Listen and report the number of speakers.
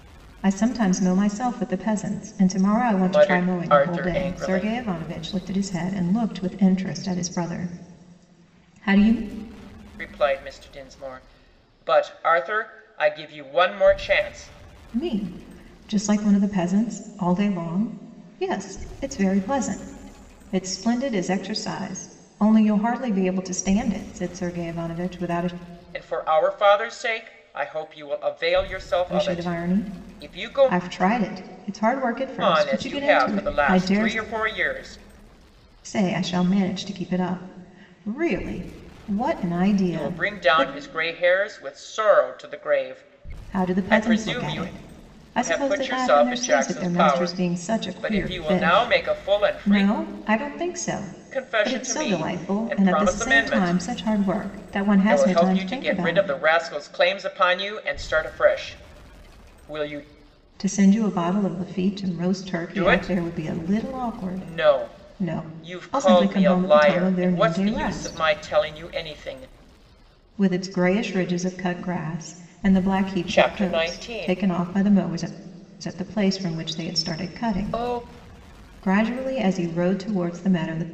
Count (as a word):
two